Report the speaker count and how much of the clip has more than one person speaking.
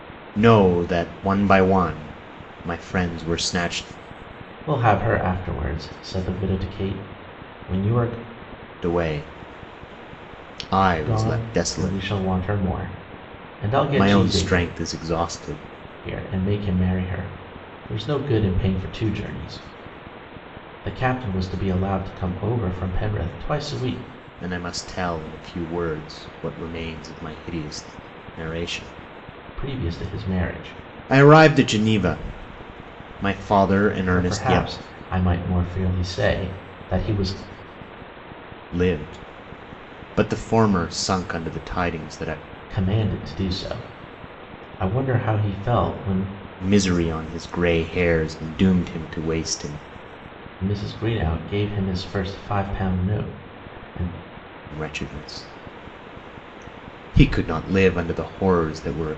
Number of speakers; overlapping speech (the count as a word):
two, about 4%